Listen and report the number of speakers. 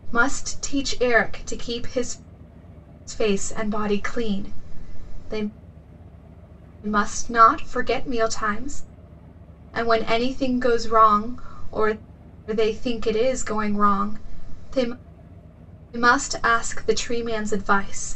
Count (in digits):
1